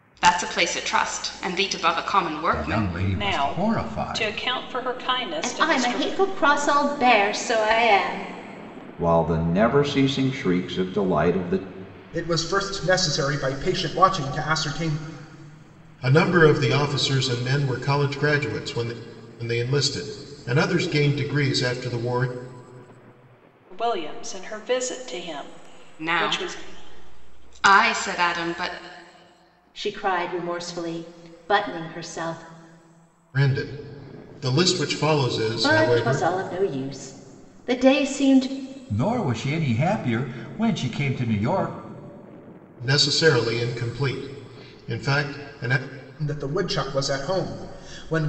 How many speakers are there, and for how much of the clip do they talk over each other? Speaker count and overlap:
seven, about 8%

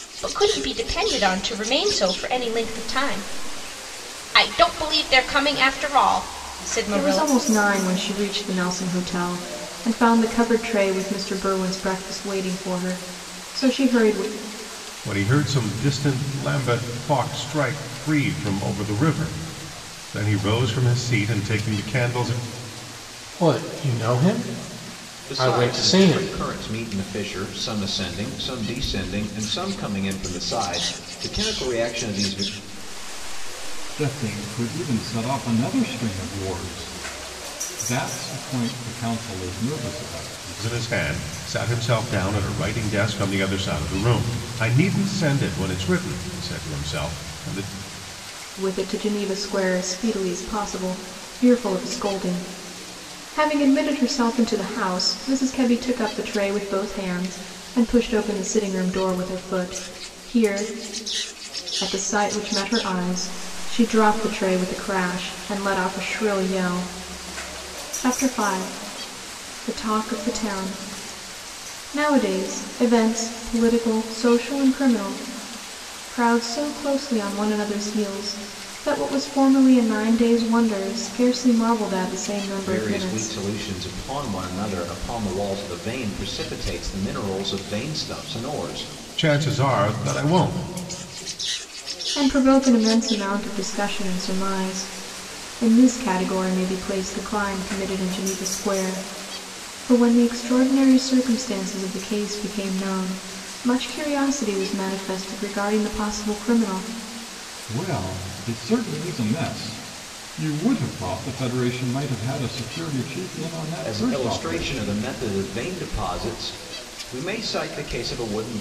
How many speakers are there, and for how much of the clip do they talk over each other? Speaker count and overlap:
six, about 3%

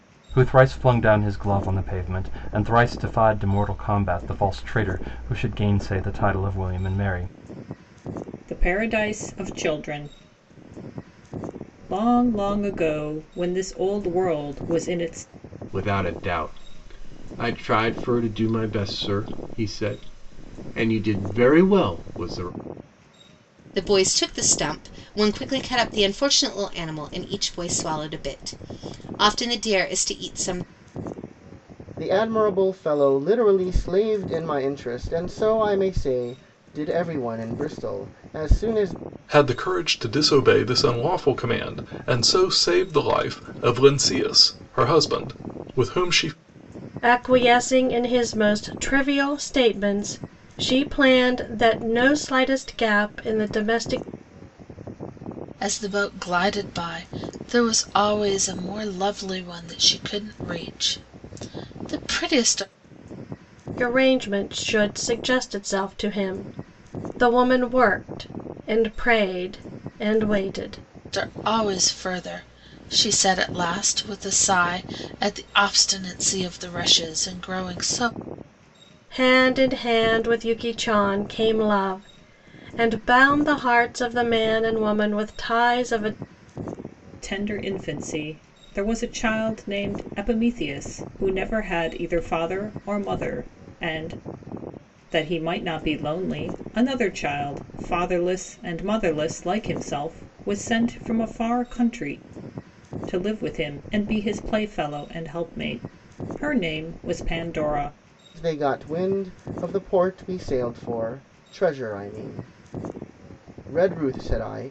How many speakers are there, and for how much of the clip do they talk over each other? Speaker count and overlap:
eight, no overlap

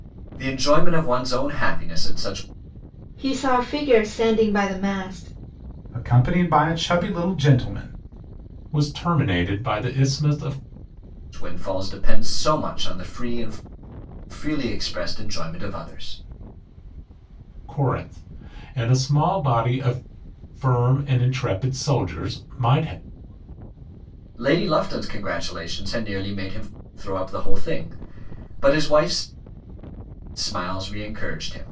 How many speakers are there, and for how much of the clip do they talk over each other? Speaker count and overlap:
four, no overlap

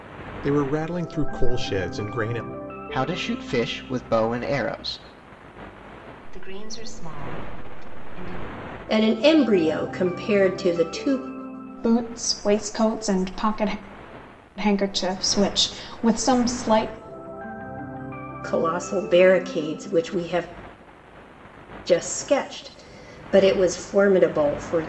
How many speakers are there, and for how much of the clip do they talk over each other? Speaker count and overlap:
five, no overlap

